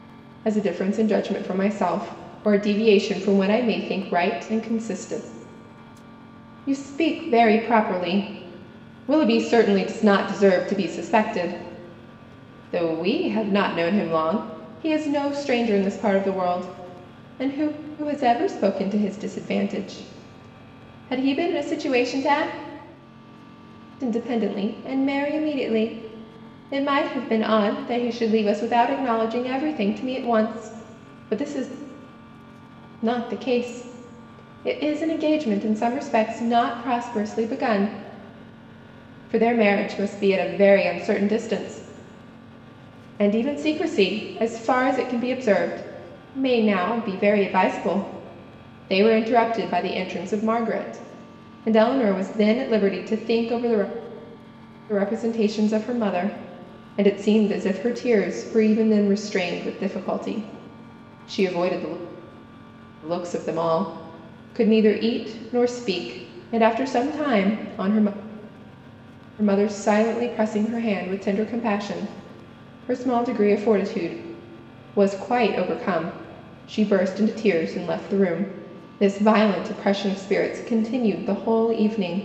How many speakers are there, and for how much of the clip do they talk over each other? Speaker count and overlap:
one, no overlap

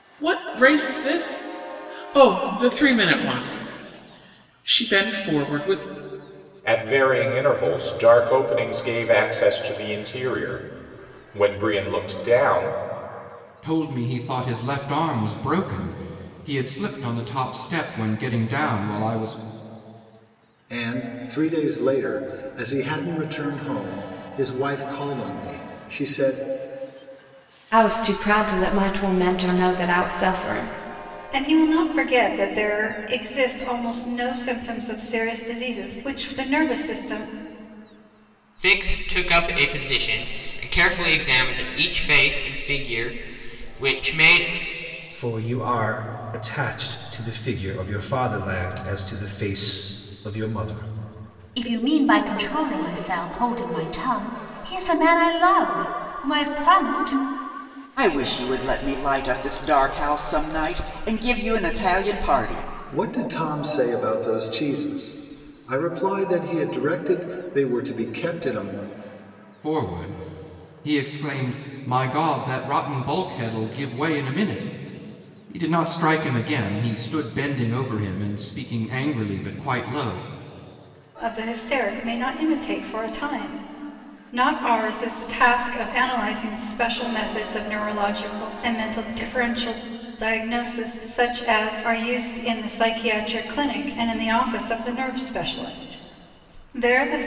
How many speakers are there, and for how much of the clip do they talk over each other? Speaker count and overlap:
ten, no overlap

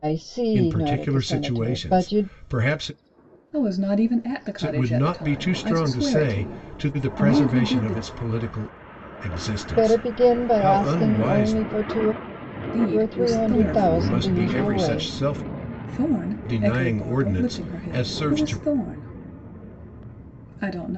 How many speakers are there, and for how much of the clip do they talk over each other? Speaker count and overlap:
three, about 56%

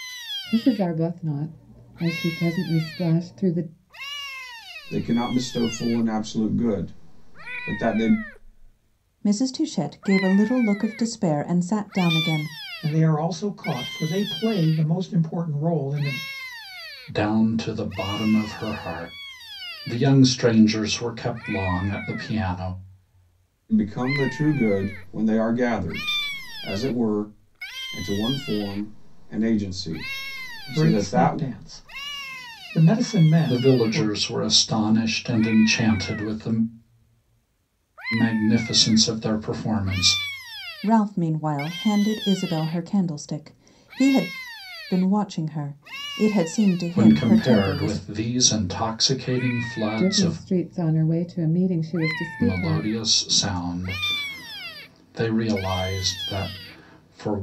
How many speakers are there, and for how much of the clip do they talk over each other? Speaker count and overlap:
five, about 6%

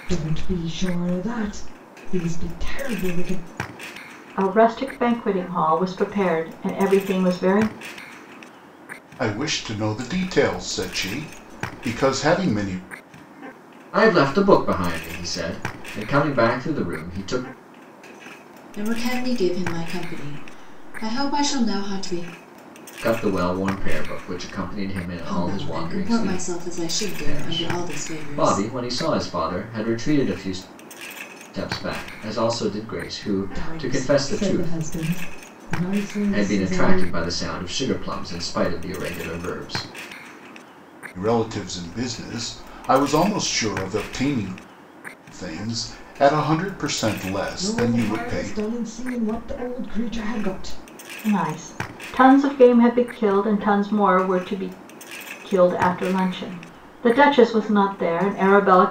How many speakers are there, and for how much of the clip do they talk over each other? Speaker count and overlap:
five, about 10%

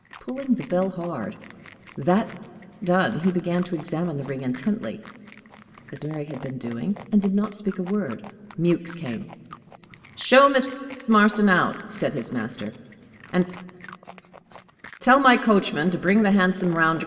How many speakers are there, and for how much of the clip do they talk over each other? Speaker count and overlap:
one, no overlap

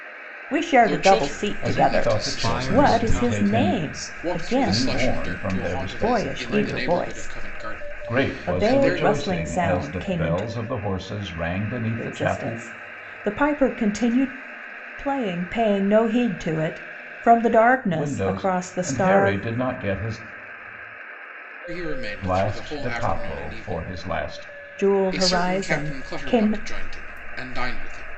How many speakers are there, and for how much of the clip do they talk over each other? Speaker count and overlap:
four, about 51%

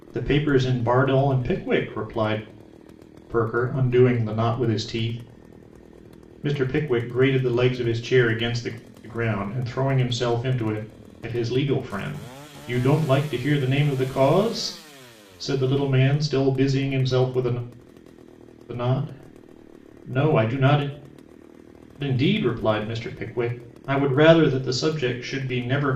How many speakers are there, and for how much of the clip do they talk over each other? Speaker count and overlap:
one, no overlap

